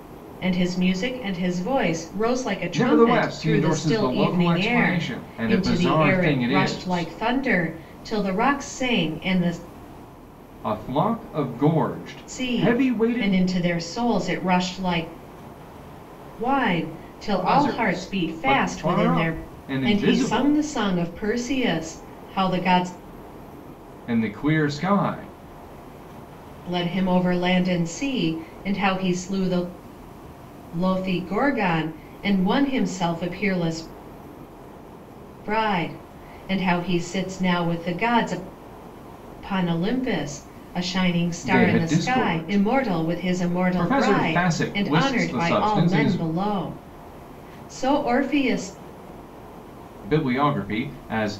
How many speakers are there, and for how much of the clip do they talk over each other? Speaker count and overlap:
two, about 24%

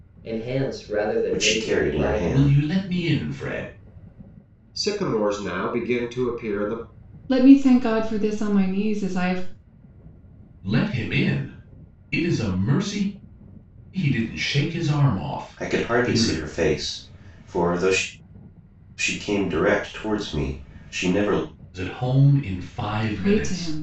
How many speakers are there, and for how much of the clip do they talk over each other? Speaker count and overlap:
five, about 12%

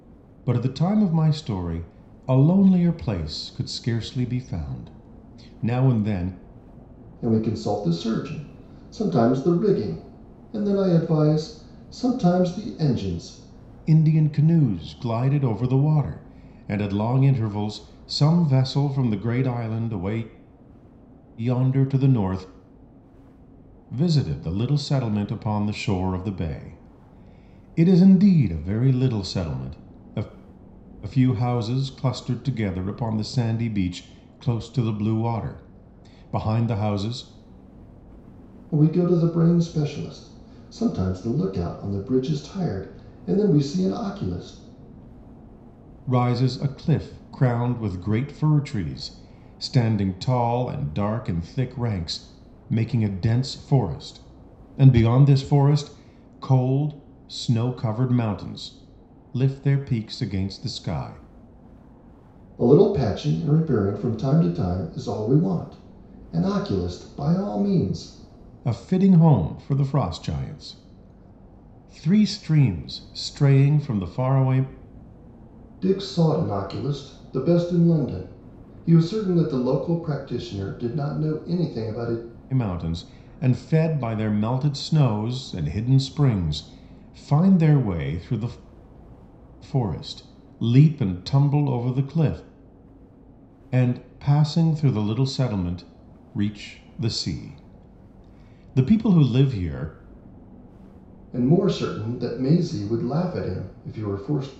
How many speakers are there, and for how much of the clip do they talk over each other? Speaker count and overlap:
two, no overlap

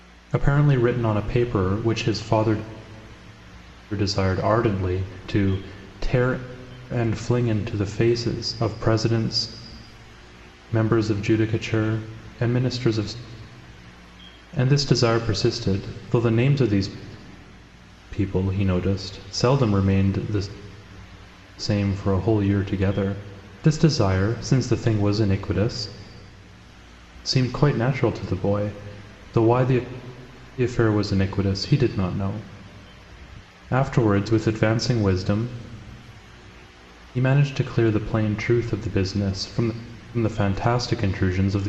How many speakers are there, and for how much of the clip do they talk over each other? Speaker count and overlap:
one, no overlap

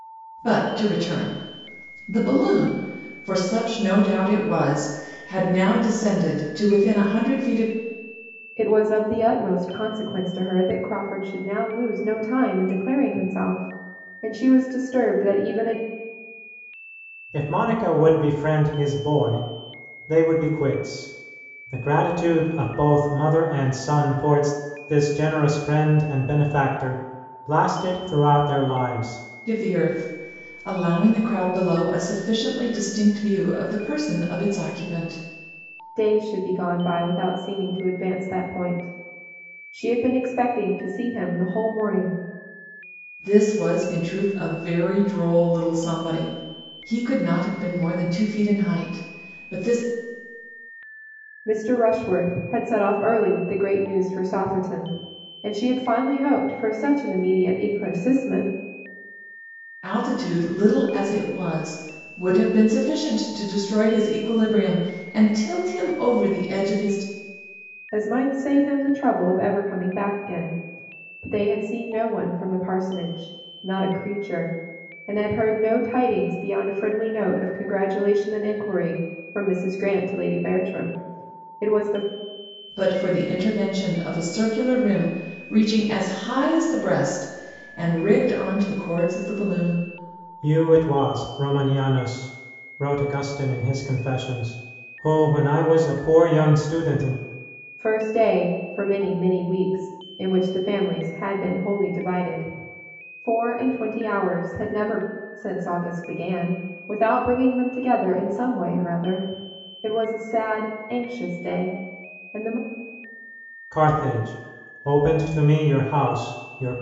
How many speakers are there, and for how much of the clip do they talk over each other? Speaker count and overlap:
three, no overlap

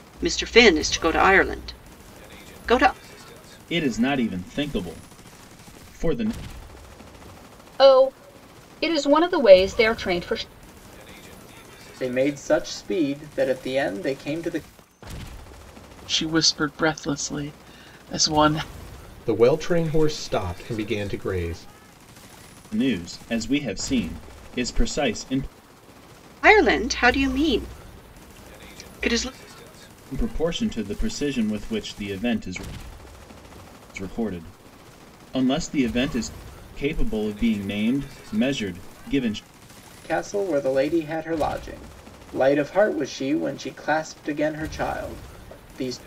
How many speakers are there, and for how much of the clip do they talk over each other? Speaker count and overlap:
six, no overlap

